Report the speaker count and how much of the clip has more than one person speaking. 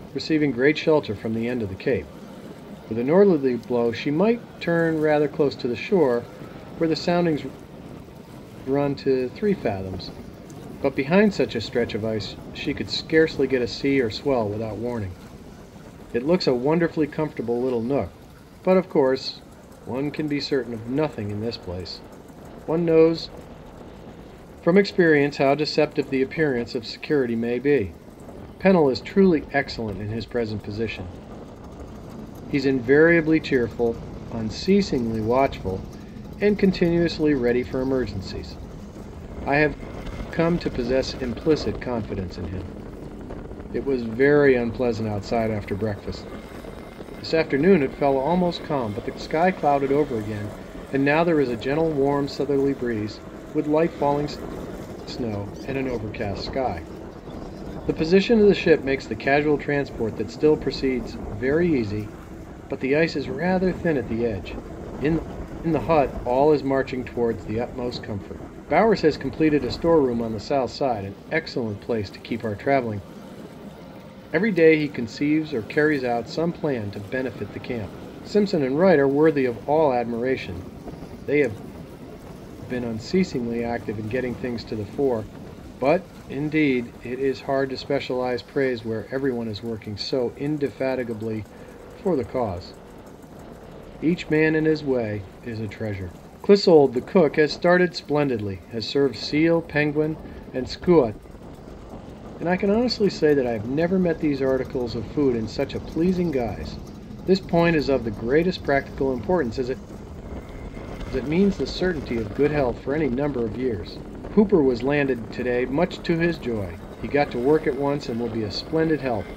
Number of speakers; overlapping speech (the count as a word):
one, no overlap